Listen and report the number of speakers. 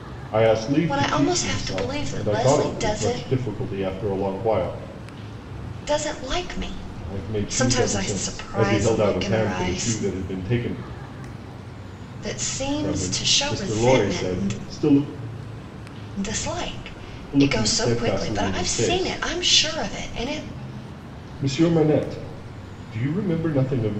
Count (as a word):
two